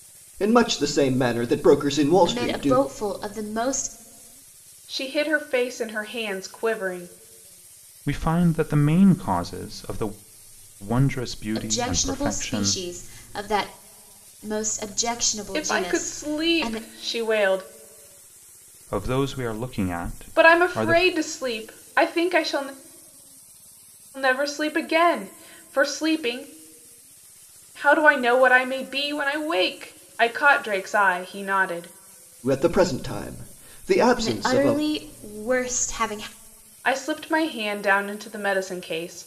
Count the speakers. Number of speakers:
four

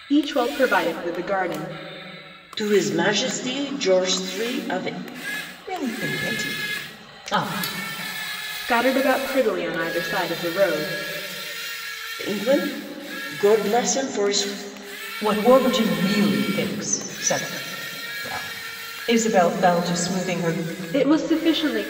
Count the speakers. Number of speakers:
three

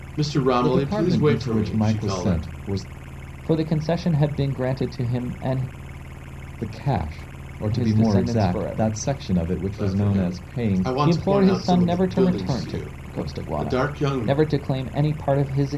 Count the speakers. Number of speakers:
three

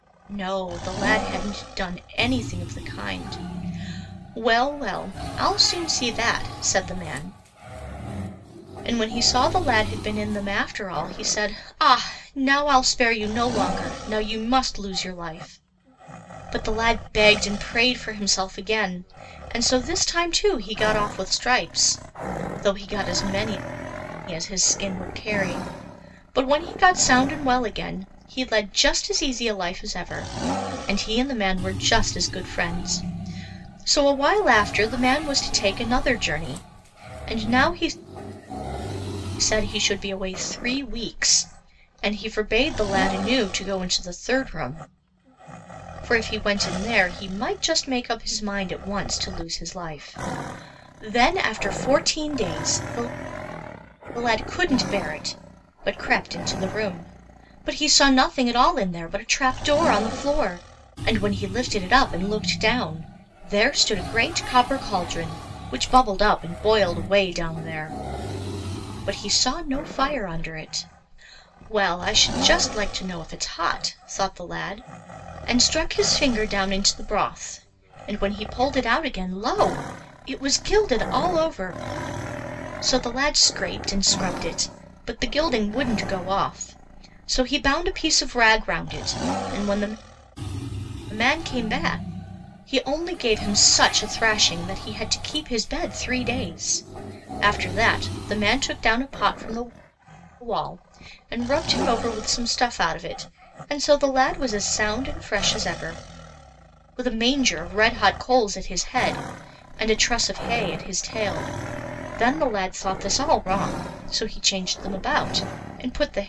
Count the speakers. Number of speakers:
one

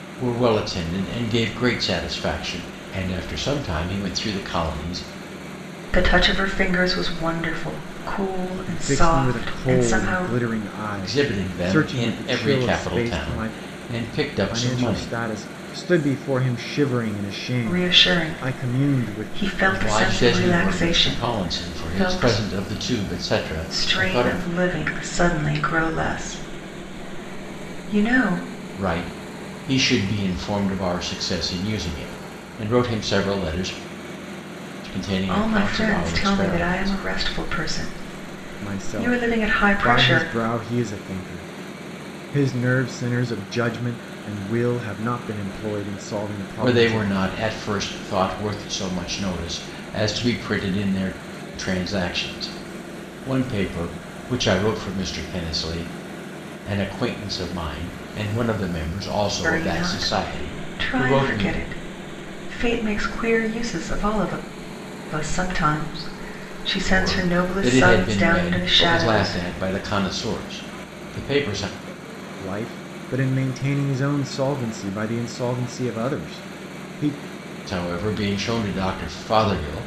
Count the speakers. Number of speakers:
three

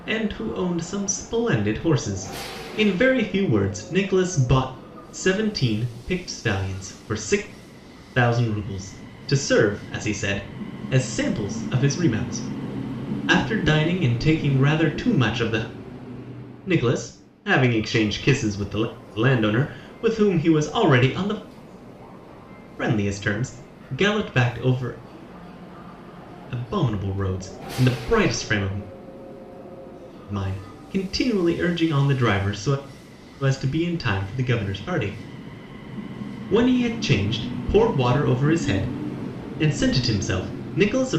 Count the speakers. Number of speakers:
one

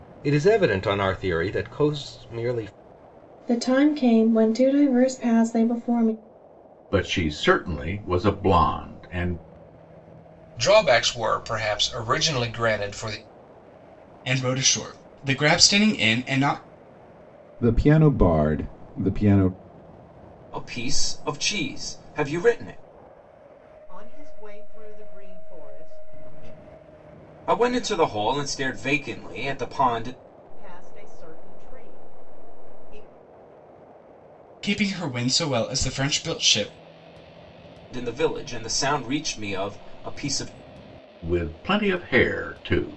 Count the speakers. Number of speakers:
eight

